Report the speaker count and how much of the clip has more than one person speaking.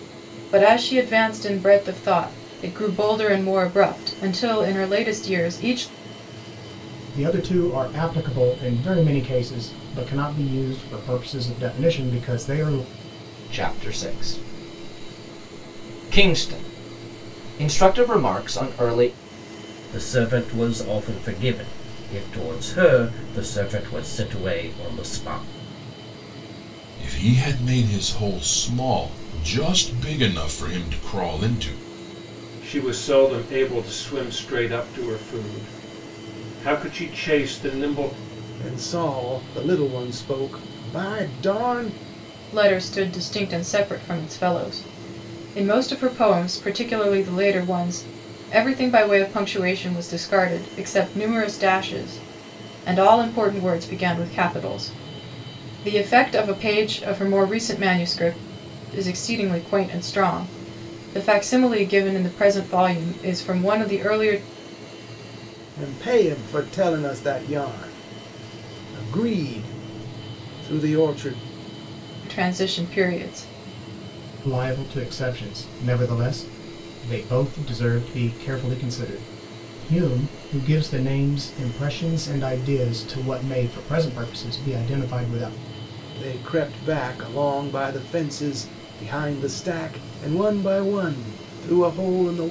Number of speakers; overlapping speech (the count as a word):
seven, no overlap